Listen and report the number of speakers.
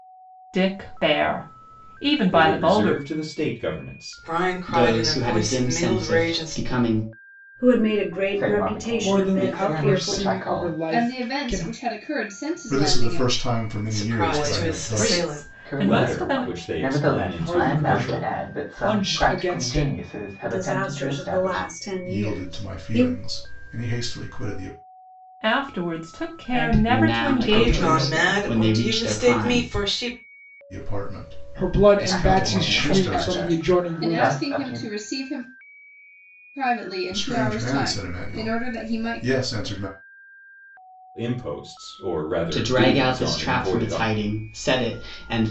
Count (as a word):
nine